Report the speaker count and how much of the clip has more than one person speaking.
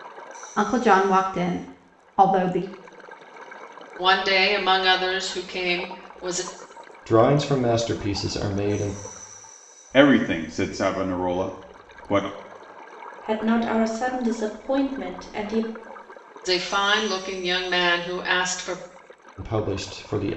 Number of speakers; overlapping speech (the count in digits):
5, no overlap